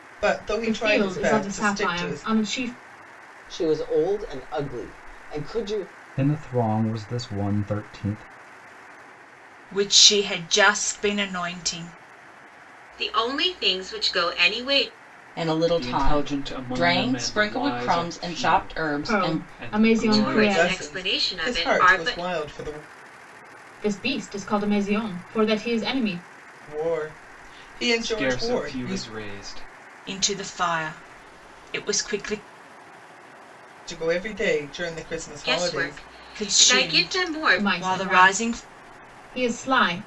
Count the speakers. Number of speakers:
8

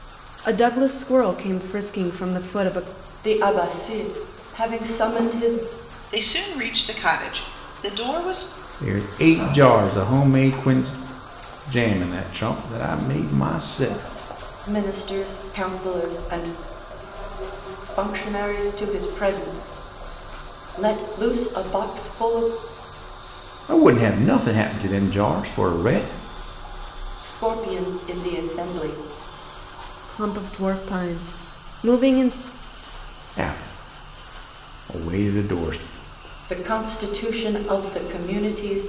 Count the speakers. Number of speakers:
4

